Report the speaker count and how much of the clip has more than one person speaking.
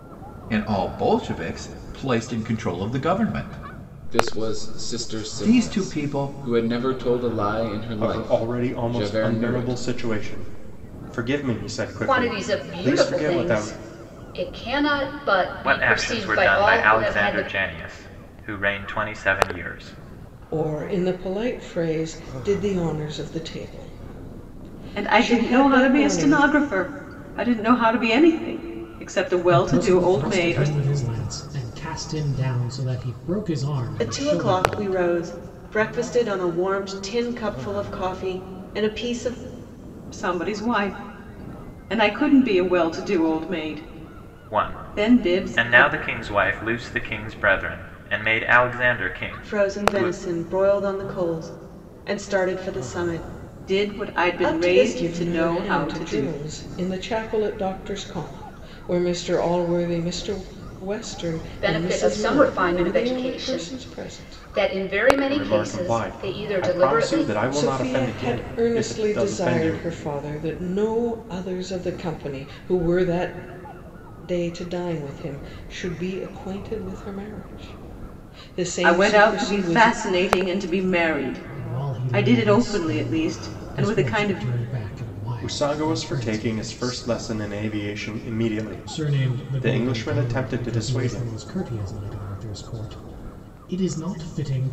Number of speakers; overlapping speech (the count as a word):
nine, about 34%